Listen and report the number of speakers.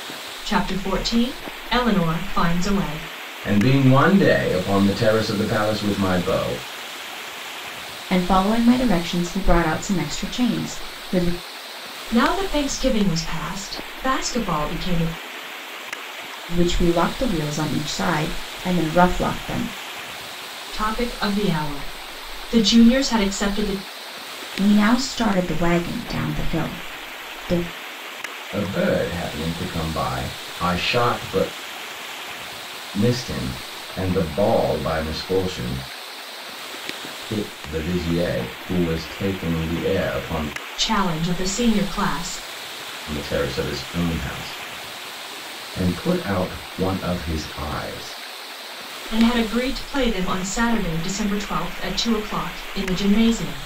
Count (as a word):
three